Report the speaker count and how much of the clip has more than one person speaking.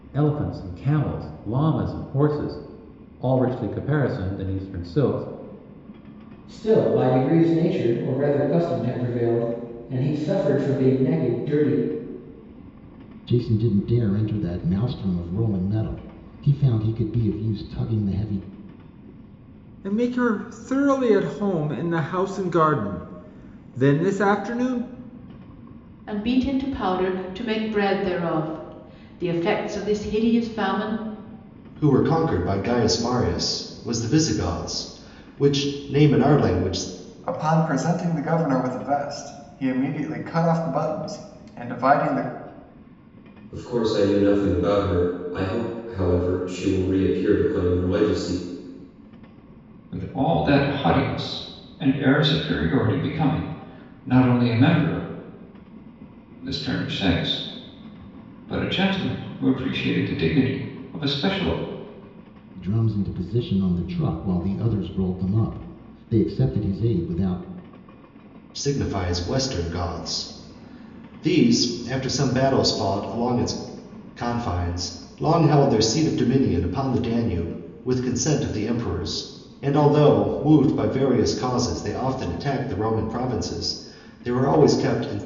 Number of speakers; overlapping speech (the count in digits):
9, no overlap